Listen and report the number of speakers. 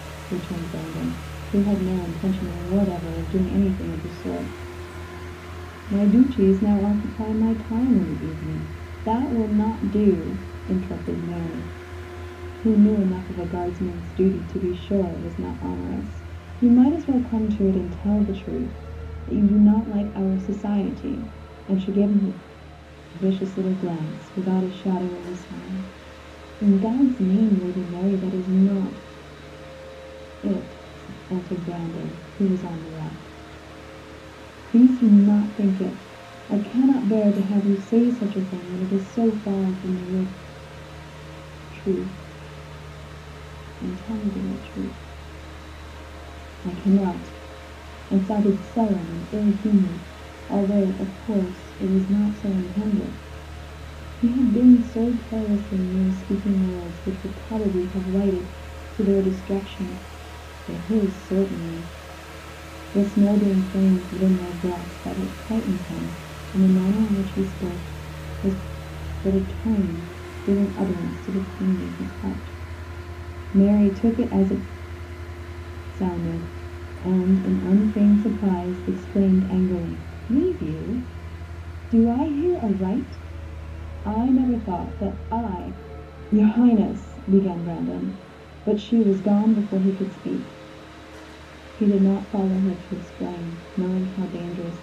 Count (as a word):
one